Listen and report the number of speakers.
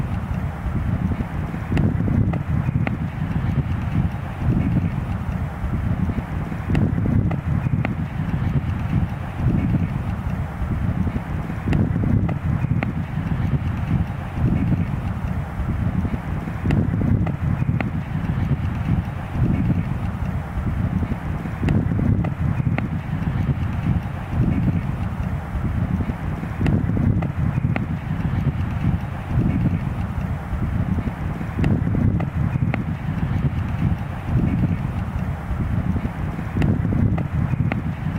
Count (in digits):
0